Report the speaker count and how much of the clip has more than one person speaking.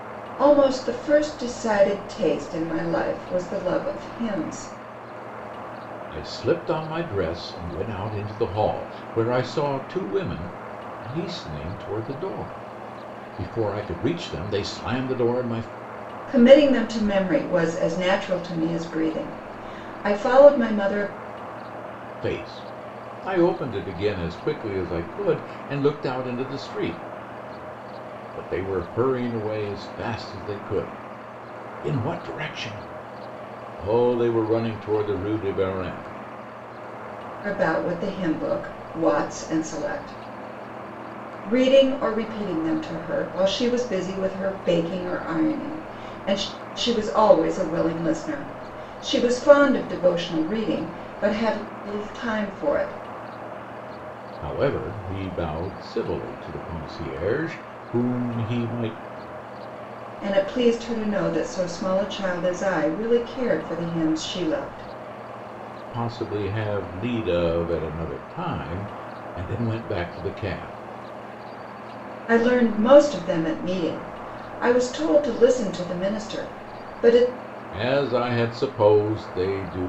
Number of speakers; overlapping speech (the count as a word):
two, no overlap